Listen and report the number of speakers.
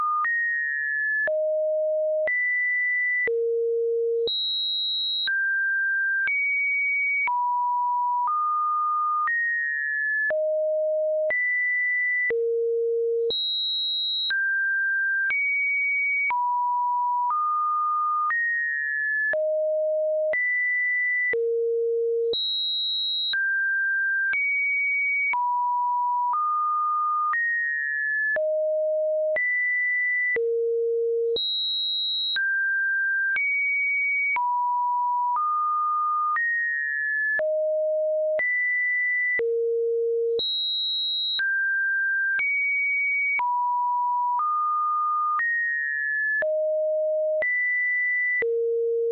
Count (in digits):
0